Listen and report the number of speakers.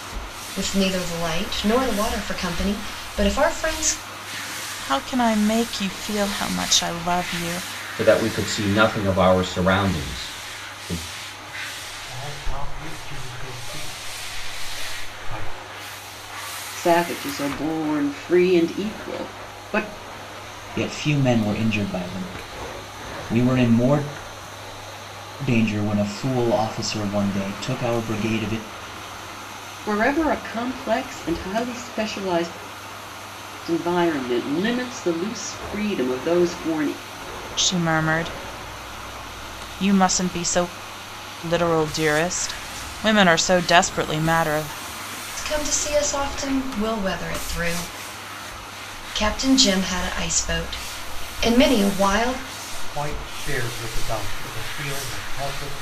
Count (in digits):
6